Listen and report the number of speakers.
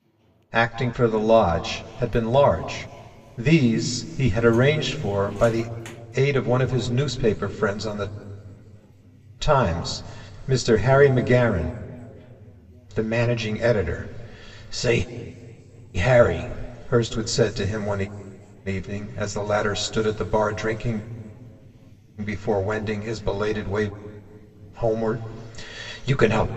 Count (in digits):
1